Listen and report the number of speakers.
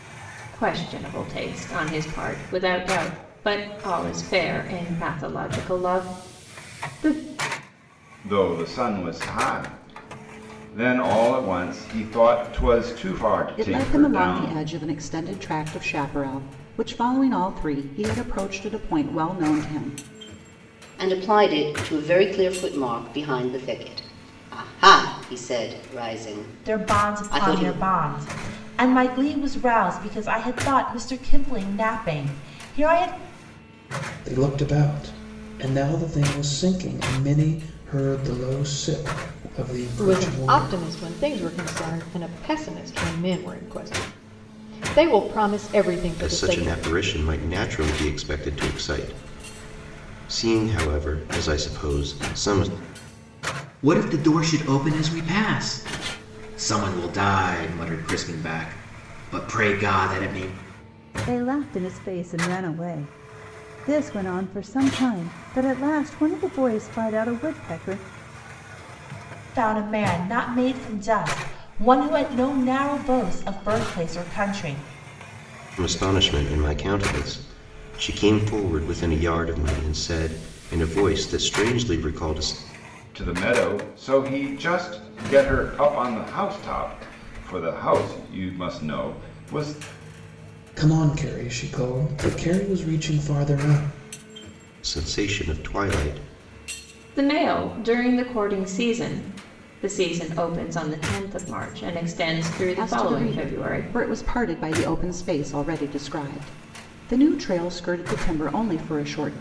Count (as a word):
ten